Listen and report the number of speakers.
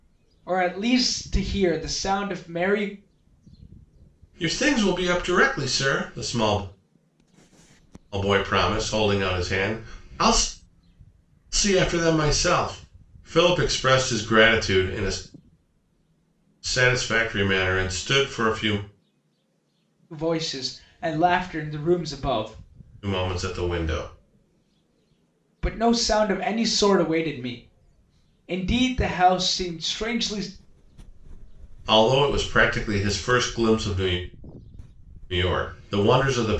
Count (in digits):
2